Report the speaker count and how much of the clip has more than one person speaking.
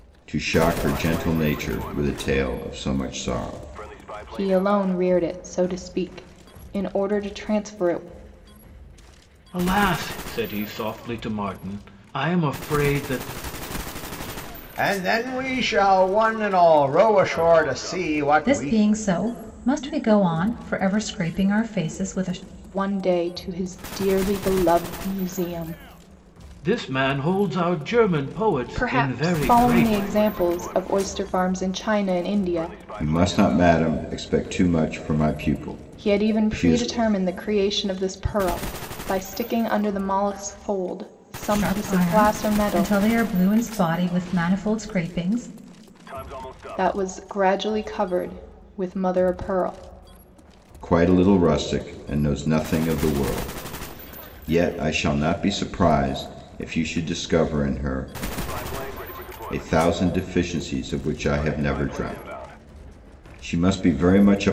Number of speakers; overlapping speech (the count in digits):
5, about 6%